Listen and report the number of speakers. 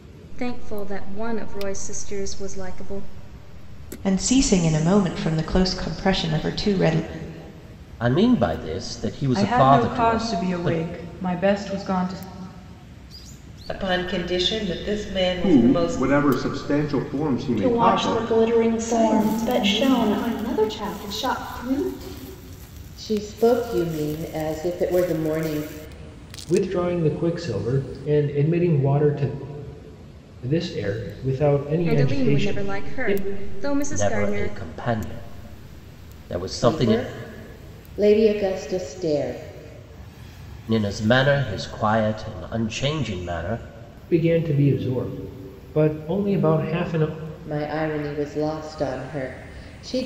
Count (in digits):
10